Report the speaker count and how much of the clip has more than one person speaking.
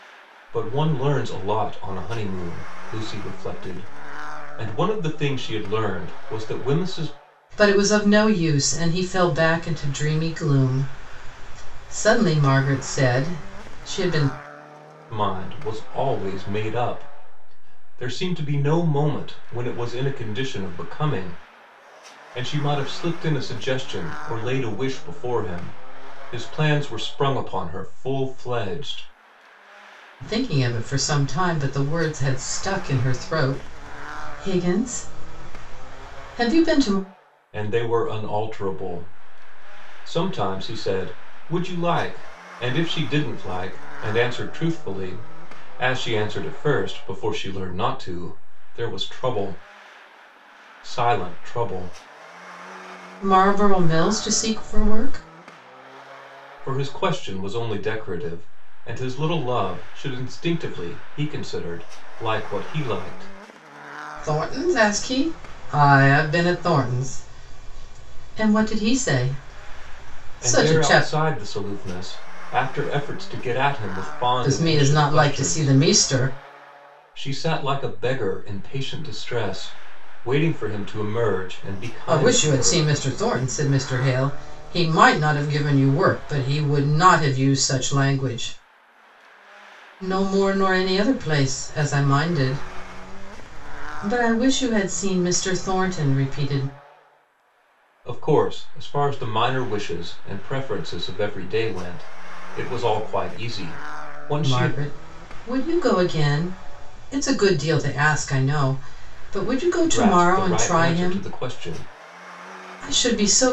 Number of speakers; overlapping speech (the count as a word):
two, about 4%